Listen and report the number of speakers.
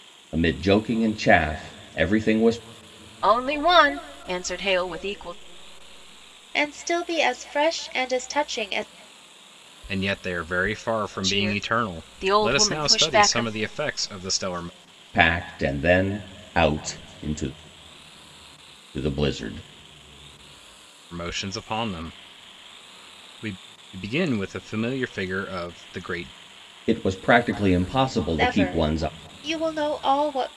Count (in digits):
4